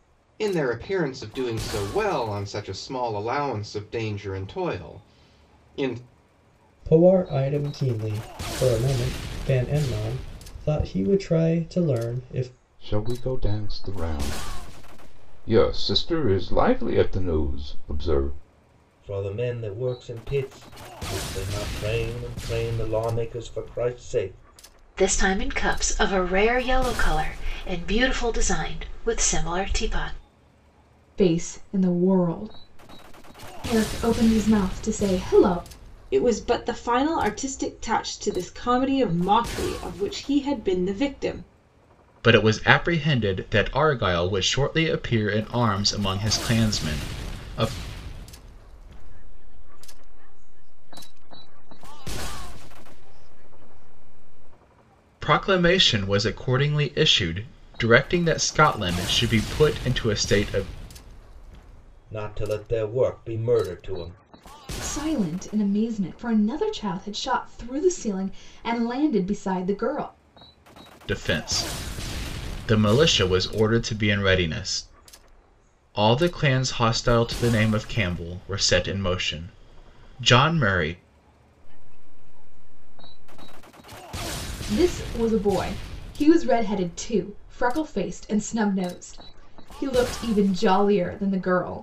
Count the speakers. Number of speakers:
9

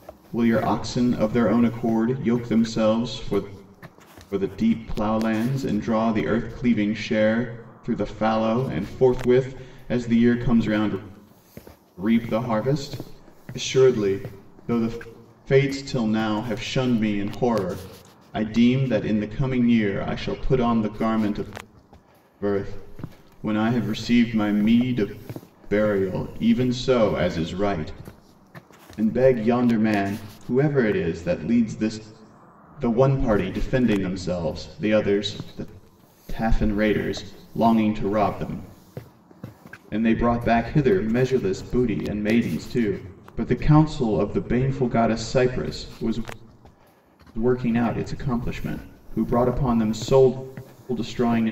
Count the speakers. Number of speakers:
1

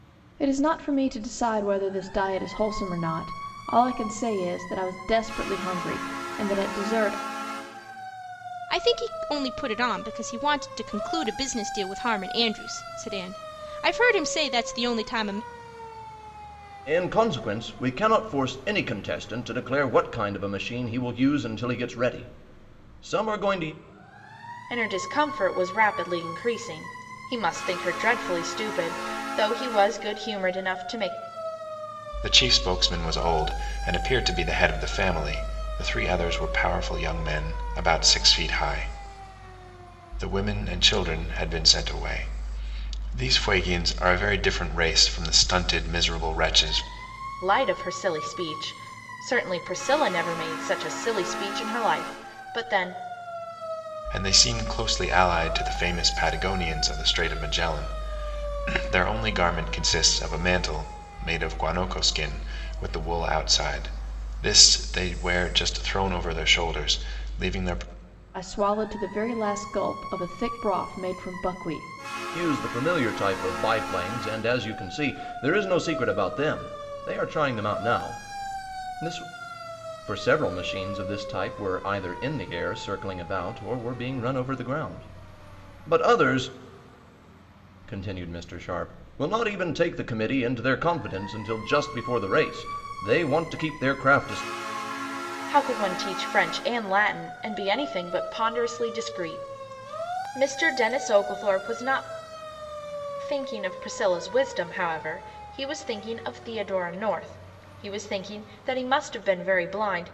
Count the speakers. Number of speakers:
5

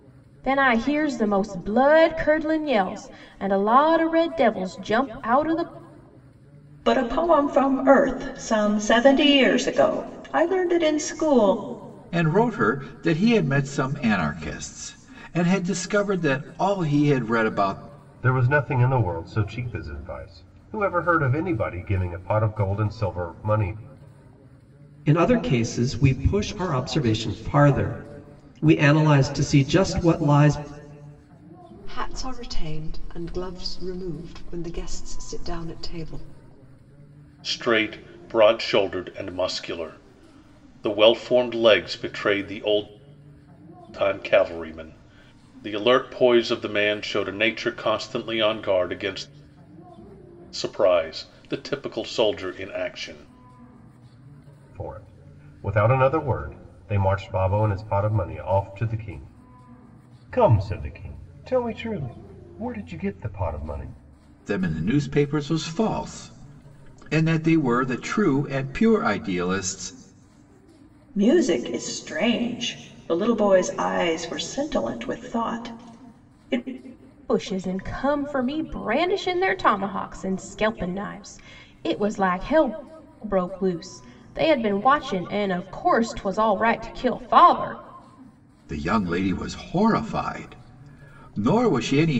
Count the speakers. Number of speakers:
7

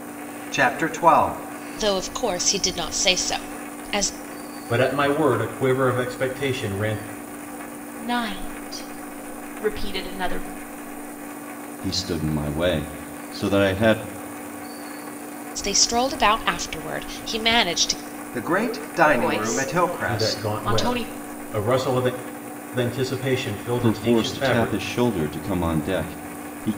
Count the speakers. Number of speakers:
5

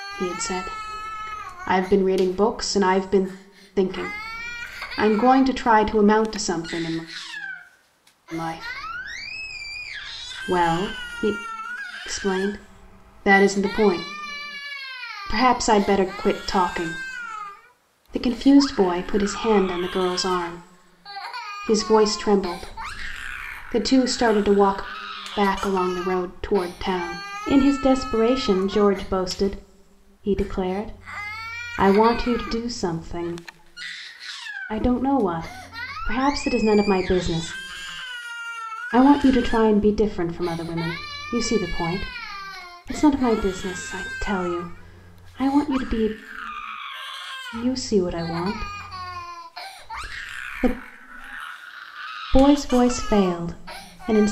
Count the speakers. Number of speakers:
1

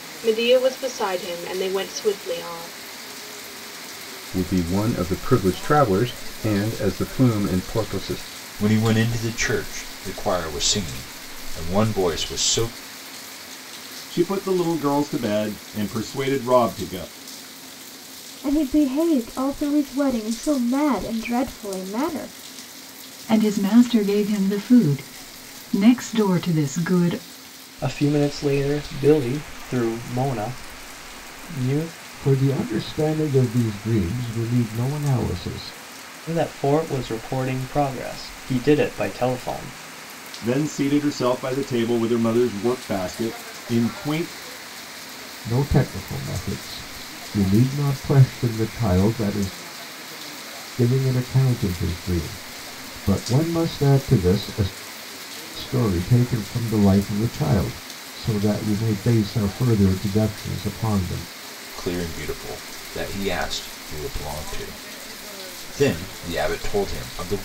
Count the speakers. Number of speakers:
8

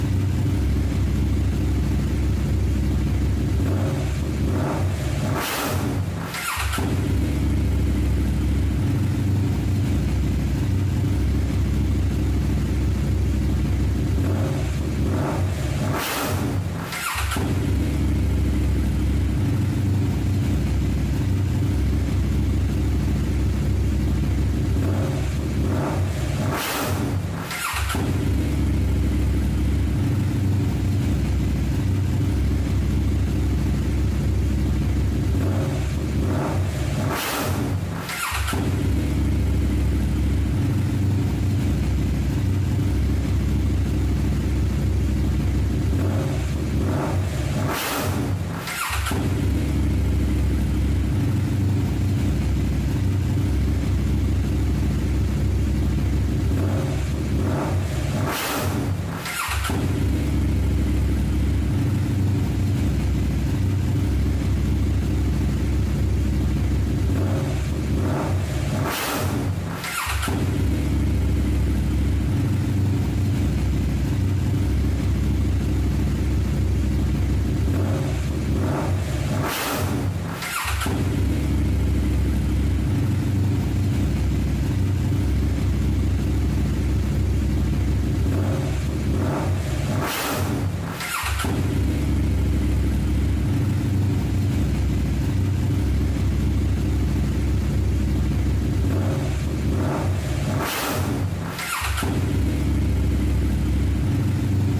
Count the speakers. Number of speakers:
0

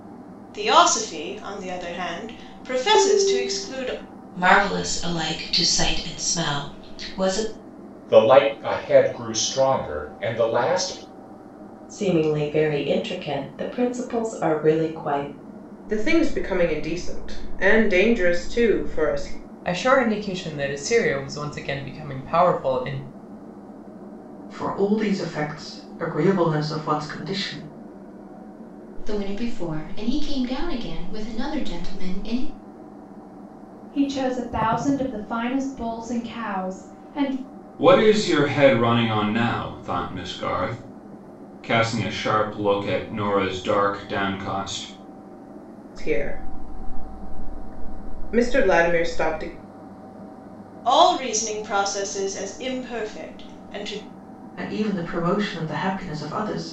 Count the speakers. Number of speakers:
10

